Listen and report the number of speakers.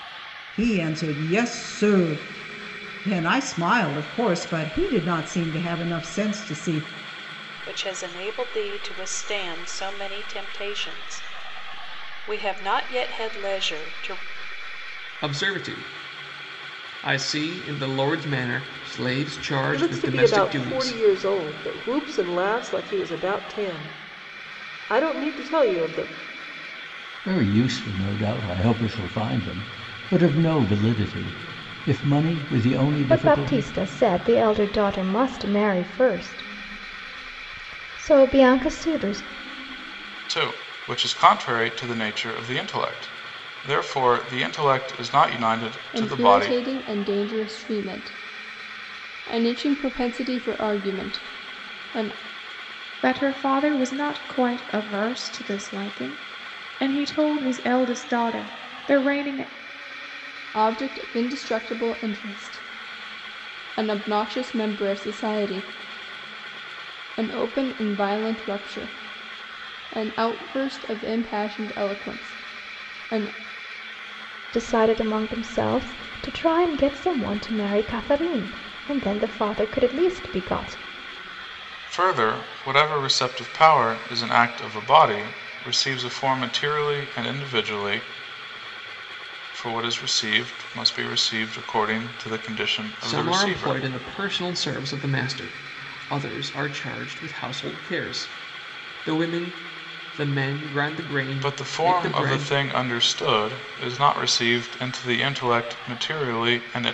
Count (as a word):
nine